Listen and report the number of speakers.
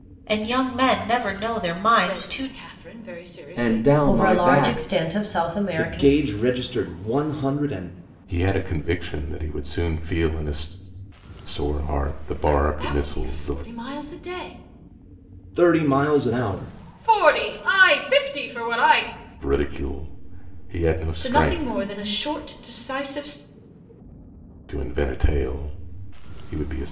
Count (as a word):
six